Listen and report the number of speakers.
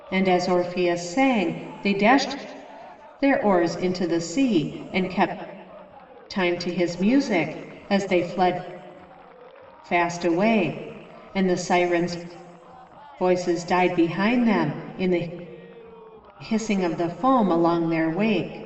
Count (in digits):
1